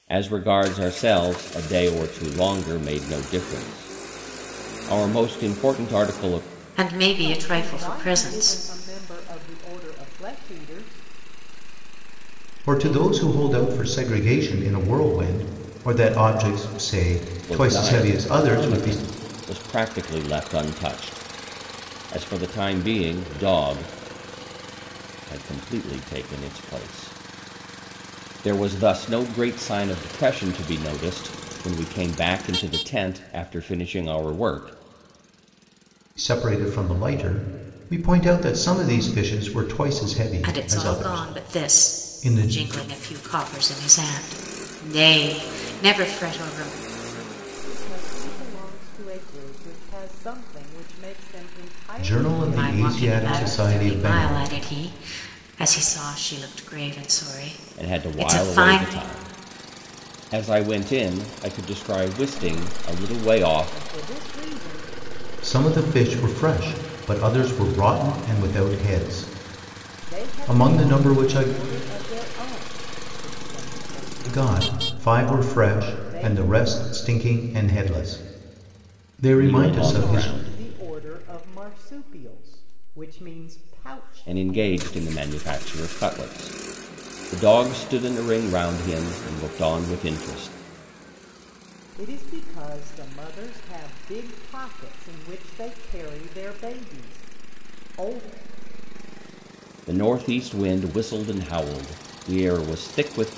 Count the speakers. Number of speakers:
four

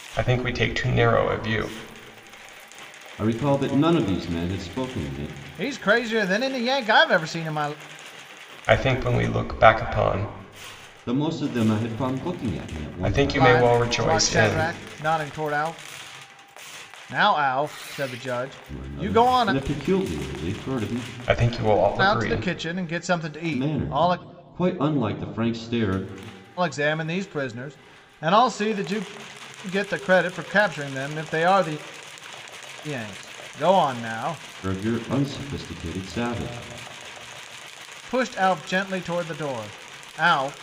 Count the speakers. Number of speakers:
three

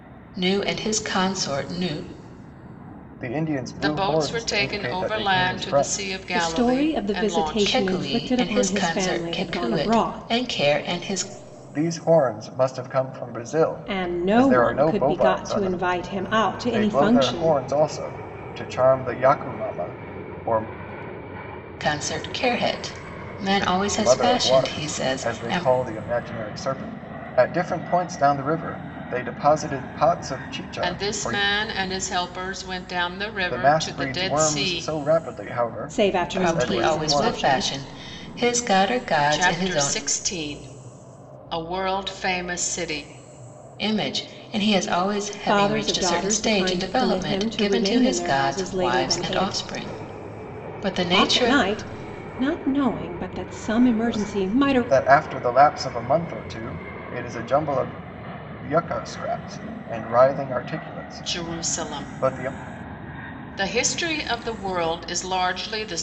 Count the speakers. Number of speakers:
four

